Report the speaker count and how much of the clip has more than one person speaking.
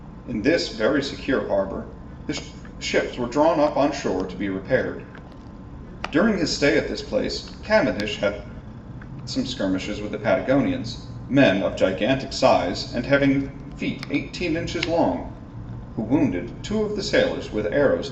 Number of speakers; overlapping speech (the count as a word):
one, no overlap